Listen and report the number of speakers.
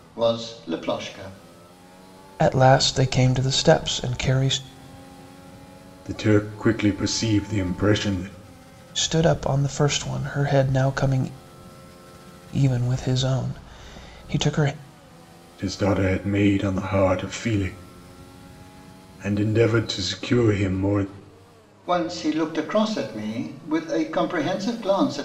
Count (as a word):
three